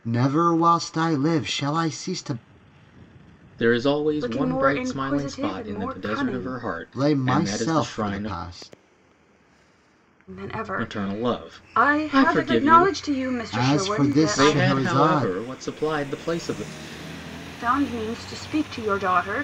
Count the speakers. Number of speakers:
3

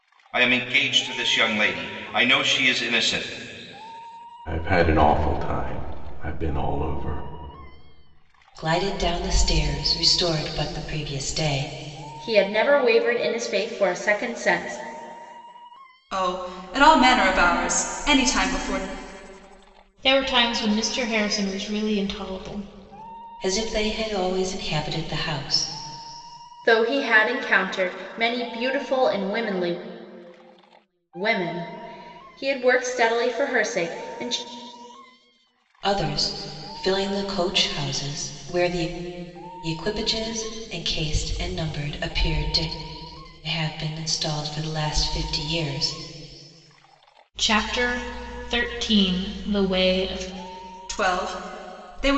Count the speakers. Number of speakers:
6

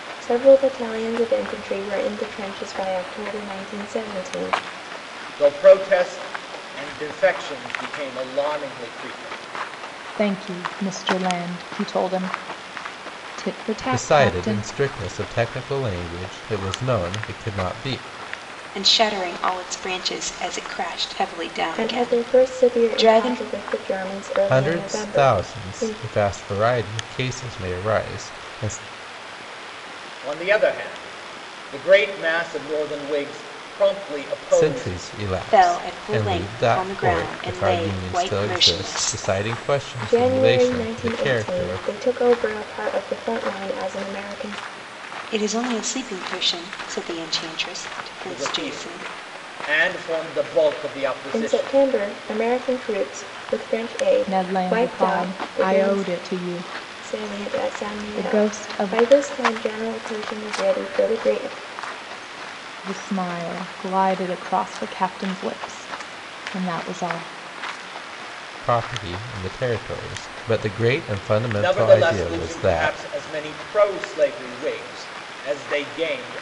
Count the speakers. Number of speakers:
5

